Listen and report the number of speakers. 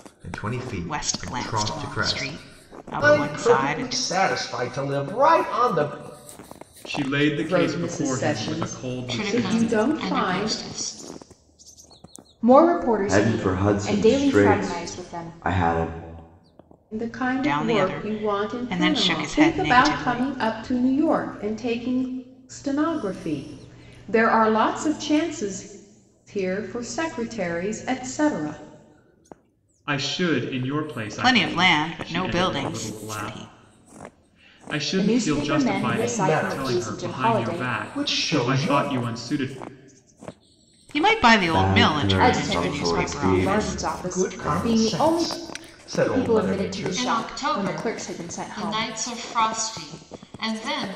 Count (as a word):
eight